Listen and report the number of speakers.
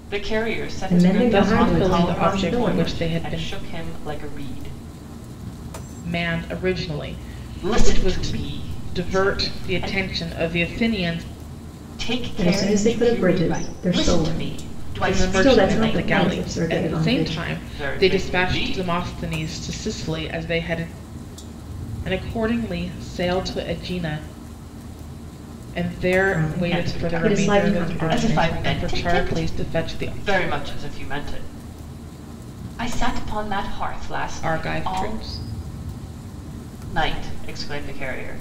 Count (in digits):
3